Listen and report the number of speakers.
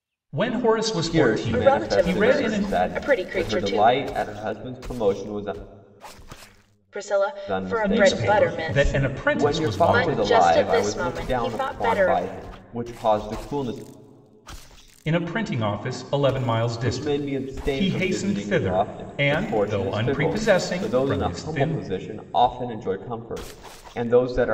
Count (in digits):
3